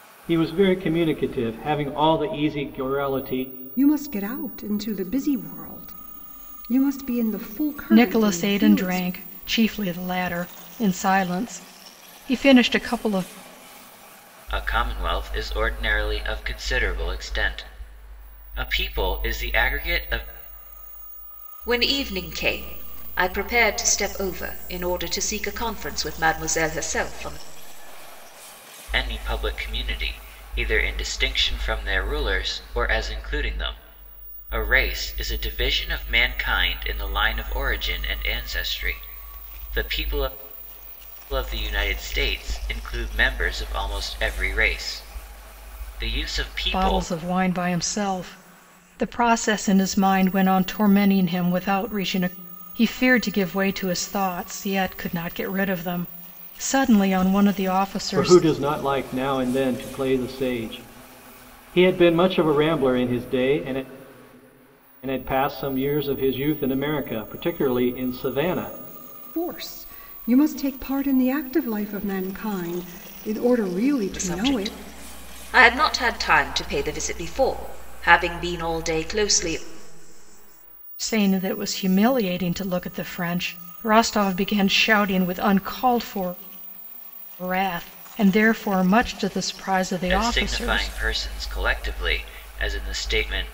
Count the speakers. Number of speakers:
5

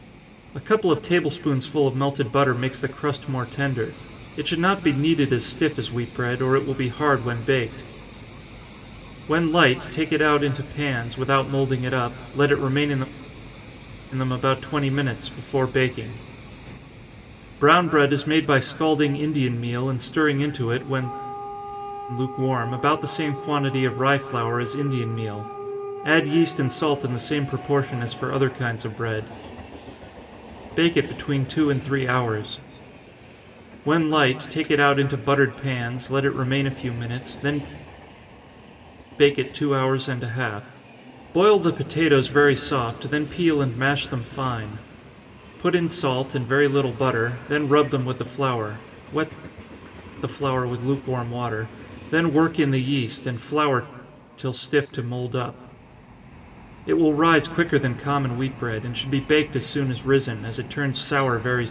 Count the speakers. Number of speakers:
1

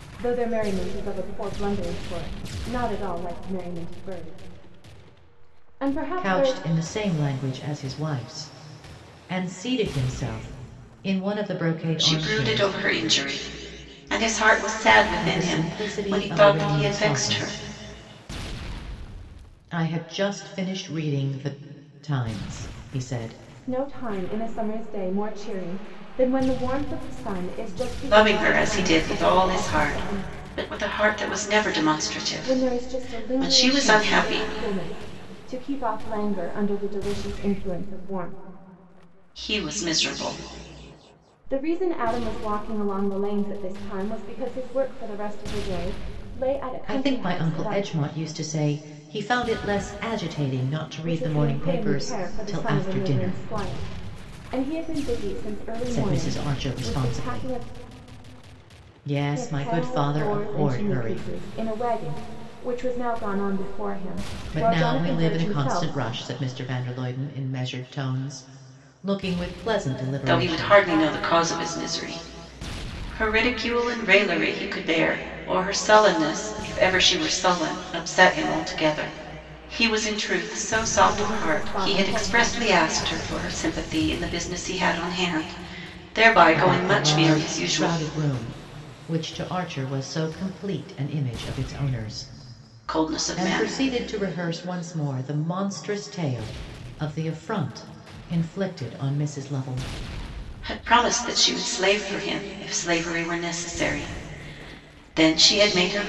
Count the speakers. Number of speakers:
3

